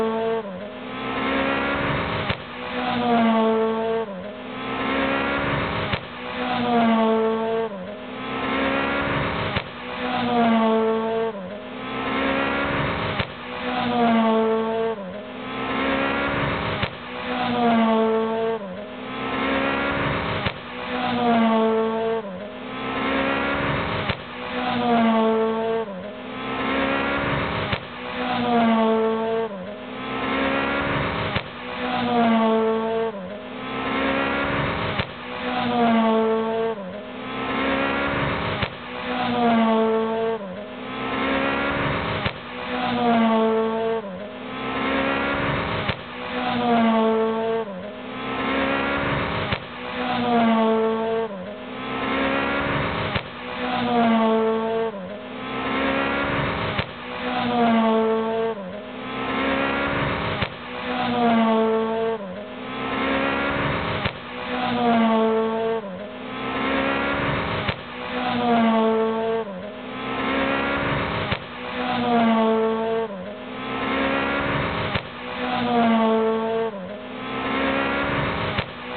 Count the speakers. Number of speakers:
0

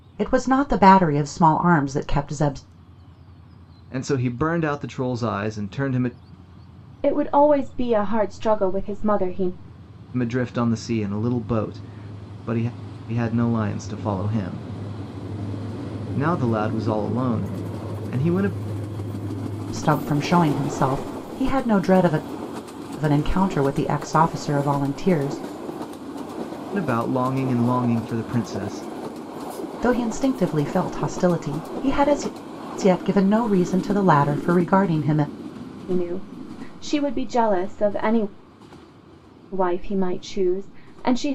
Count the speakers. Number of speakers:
3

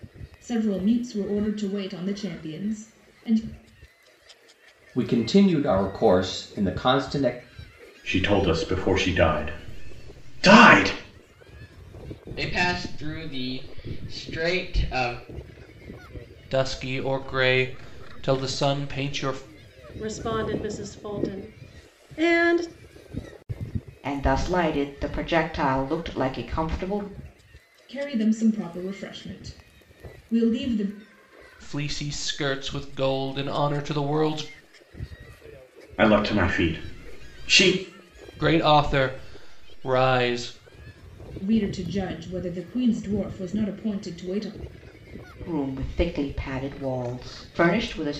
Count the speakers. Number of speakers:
7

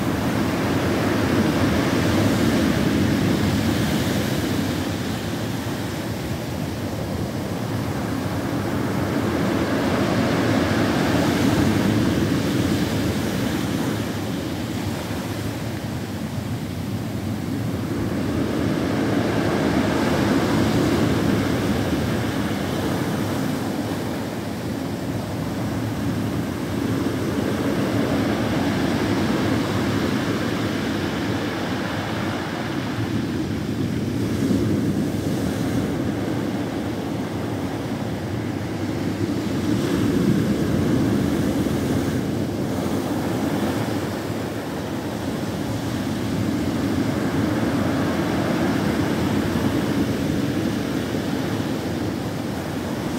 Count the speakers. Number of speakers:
0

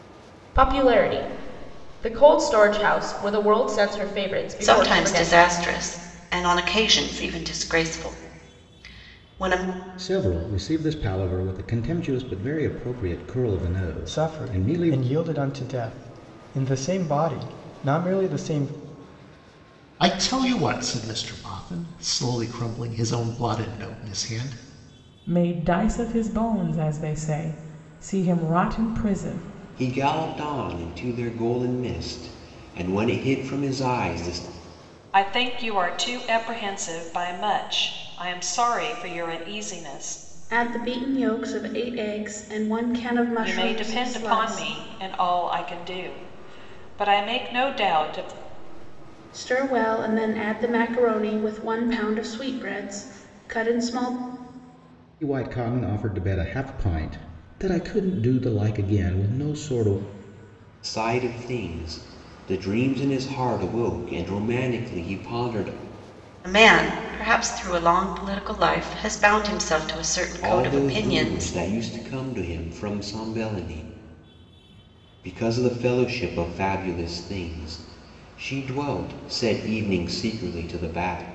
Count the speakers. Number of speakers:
9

